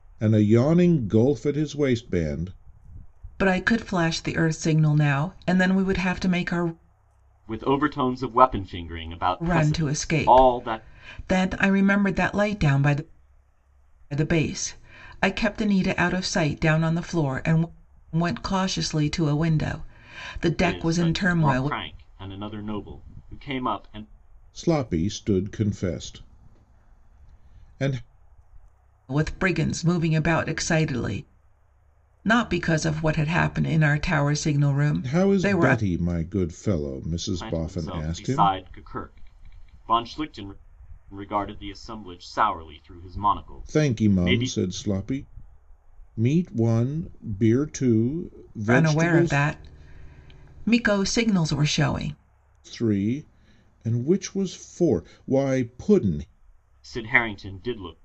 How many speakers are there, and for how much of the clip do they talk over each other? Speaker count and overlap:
three, about 11%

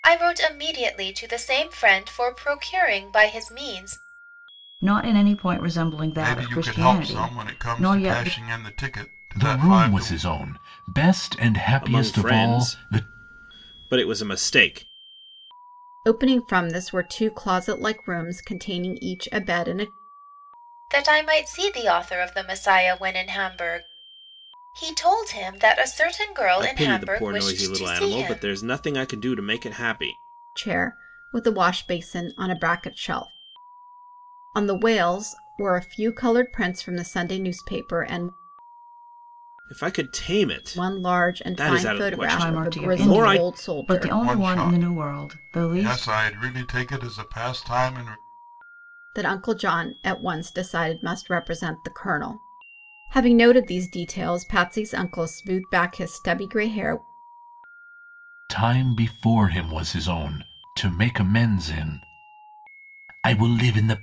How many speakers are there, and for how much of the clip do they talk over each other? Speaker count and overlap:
six, about 18%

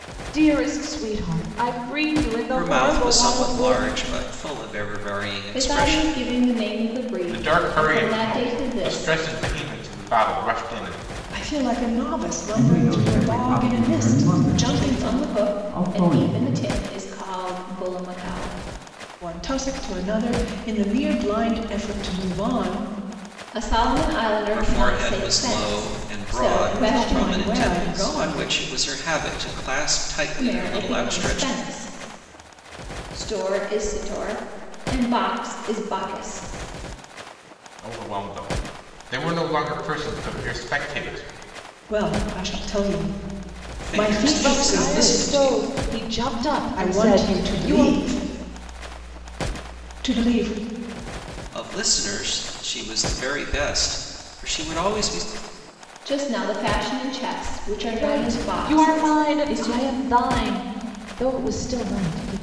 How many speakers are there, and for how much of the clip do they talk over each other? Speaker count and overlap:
six, about 29%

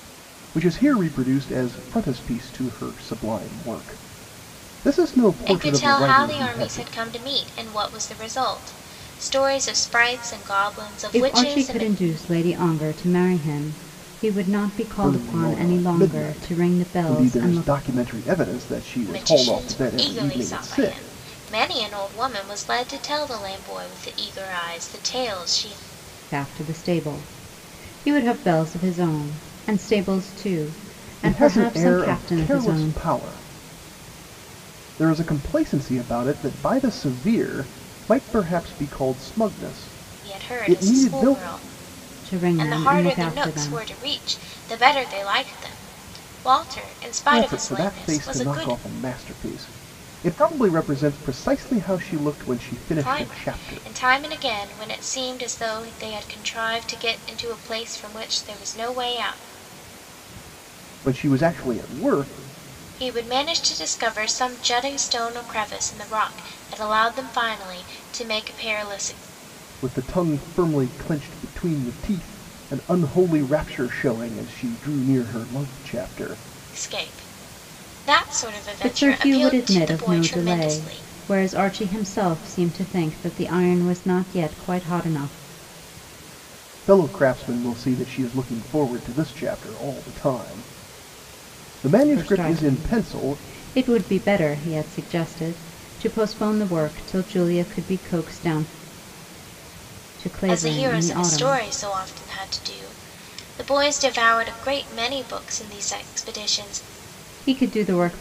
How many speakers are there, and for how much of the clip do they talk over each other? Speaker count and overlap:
three, about 17%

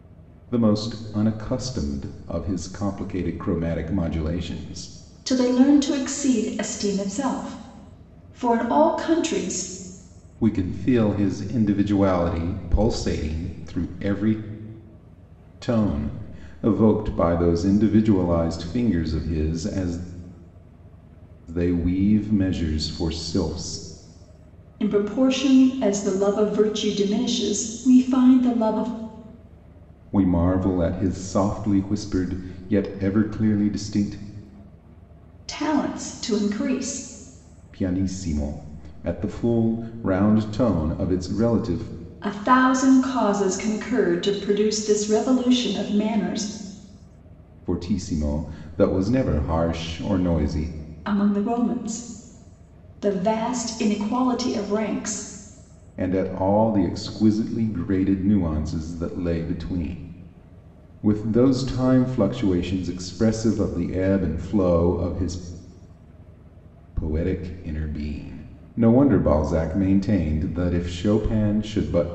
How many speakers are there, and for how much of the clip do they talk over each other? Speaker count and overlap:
two, no overlap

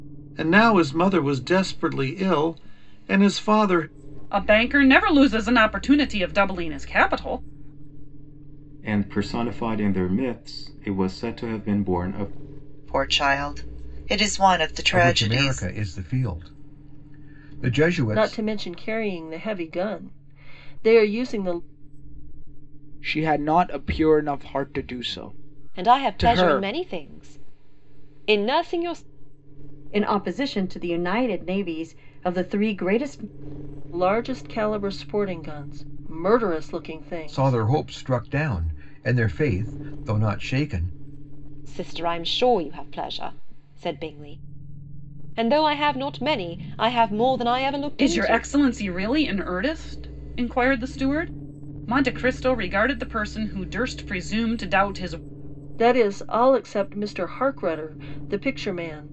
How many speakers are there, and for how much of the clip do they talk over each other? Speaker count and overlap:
nine, about 5%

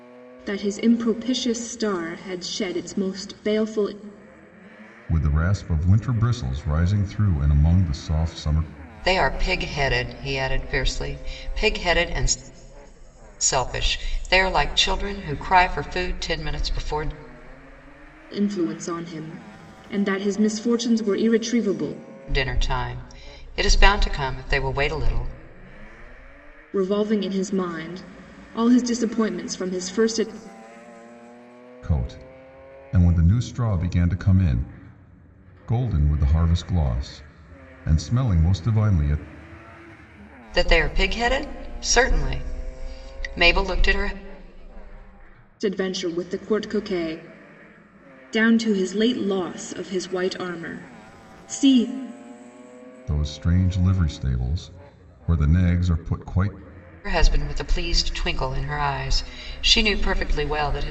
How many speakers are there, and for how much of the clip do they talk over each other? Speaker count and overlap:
three, no overlap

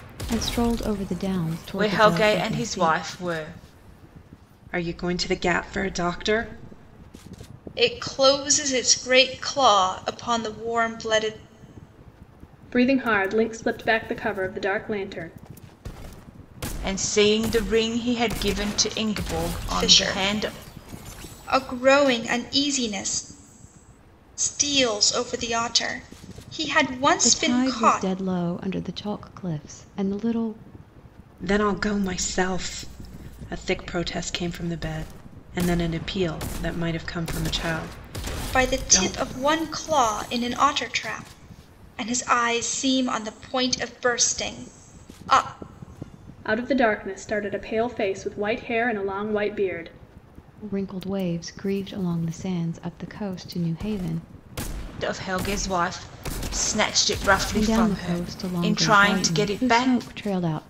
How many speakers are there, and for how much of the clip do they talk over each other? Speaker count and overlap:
five, about 10%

